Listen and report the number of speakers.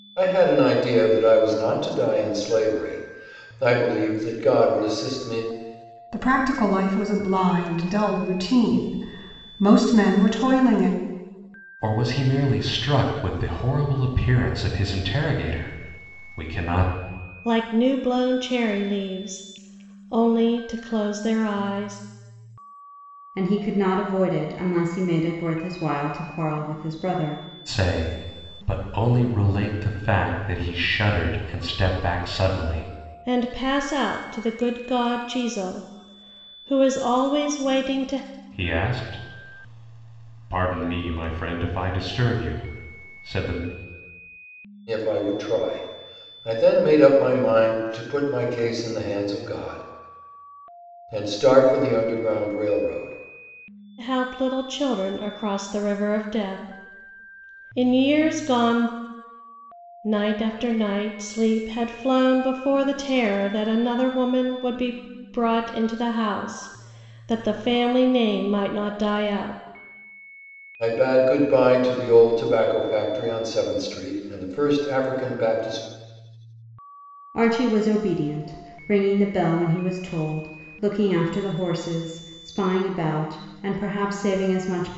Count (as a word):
five